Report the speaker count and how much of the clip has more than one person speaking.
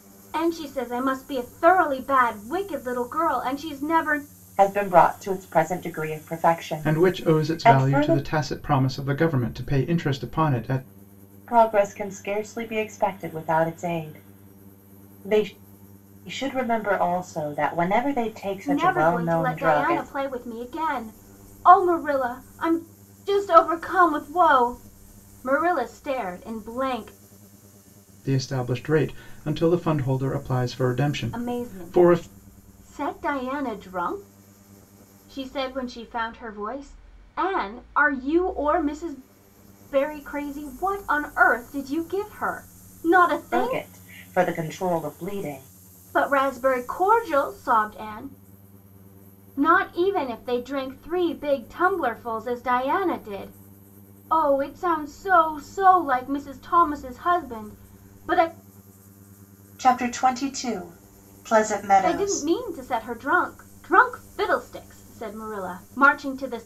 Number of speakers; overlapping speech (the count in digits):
3, about 7%